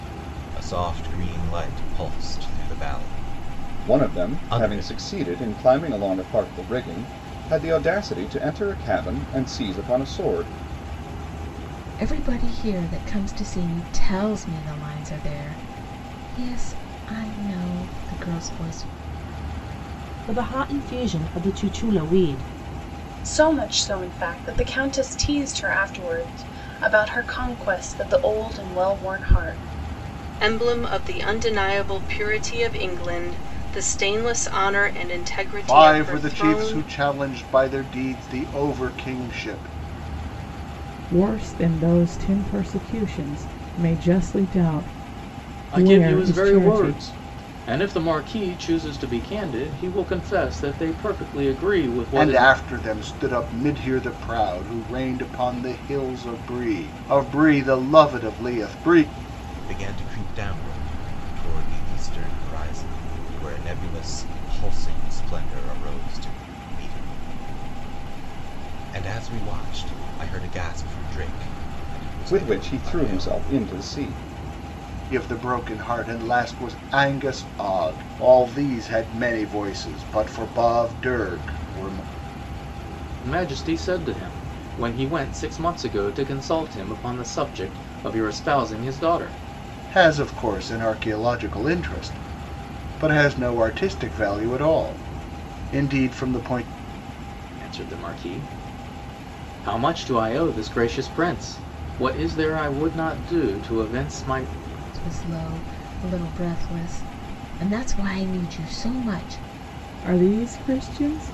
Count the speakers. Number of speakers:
9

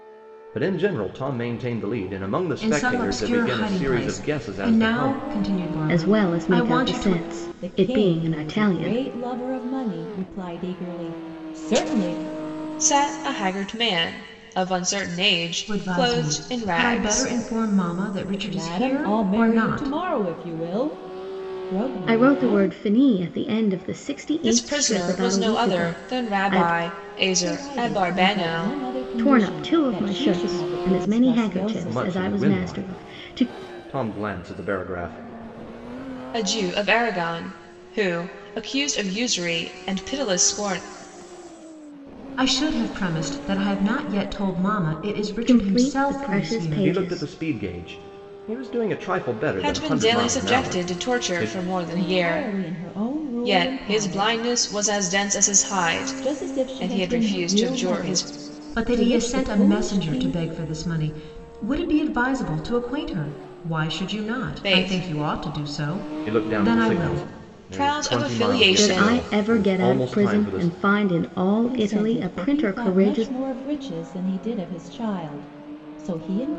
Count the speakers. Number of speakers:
5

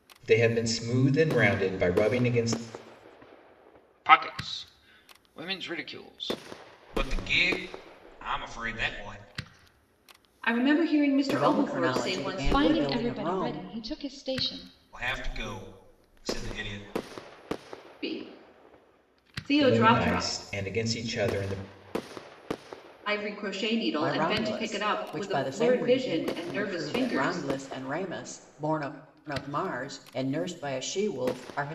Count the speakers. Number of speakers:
6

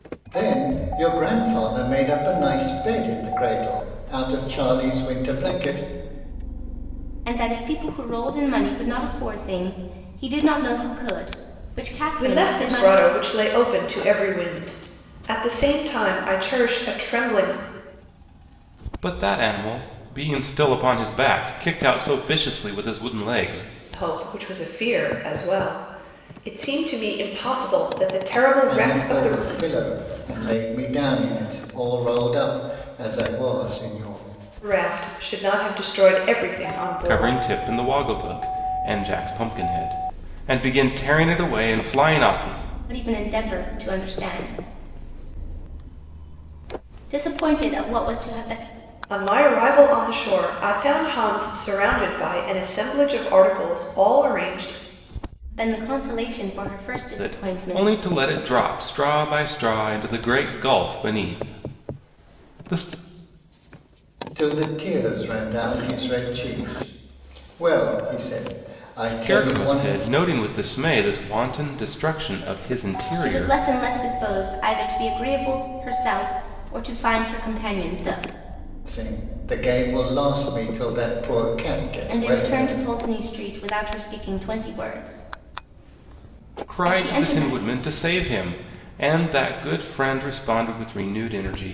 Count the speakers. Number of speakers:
4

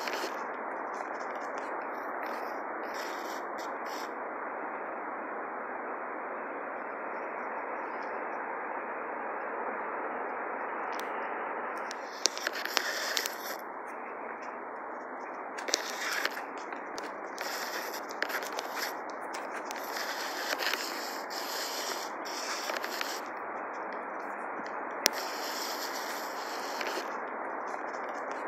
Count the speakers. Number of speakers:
0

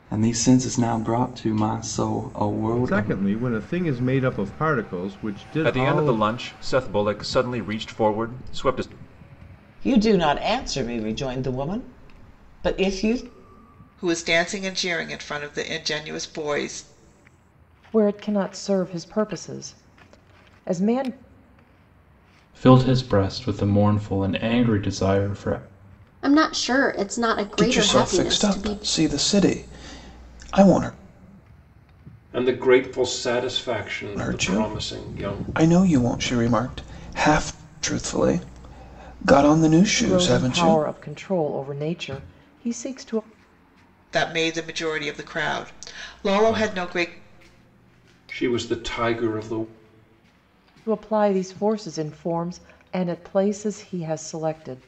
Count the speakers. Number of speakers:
10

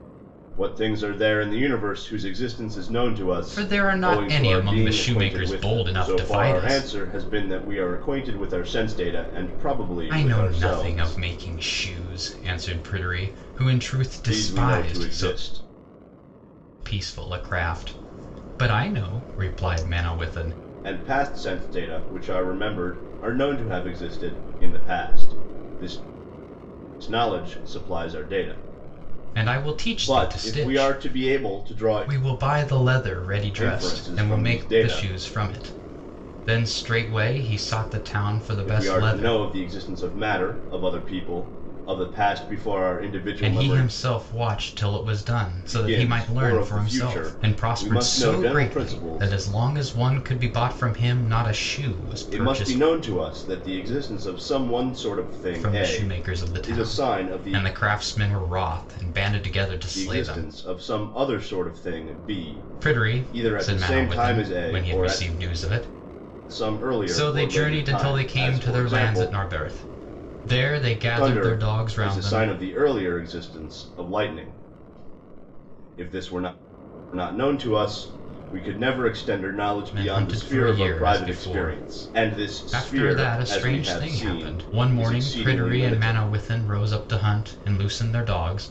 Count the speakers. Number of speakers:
2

